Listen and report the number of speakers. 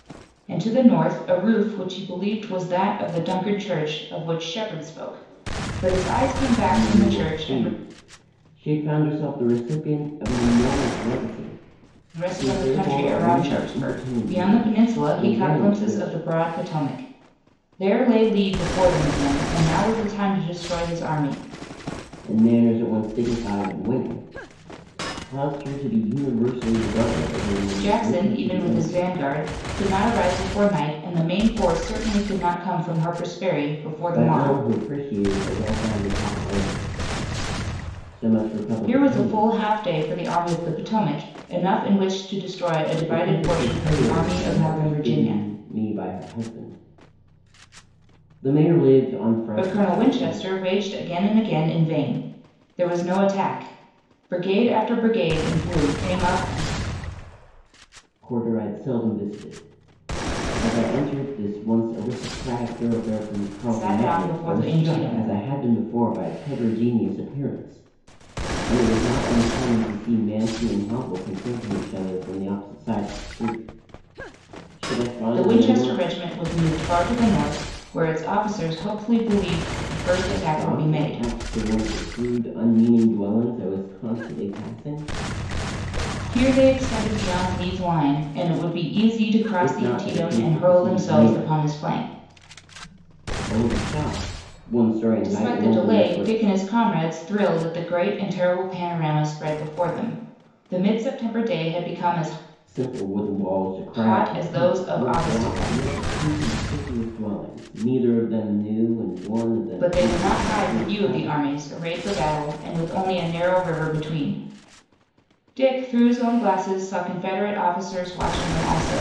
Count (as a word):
two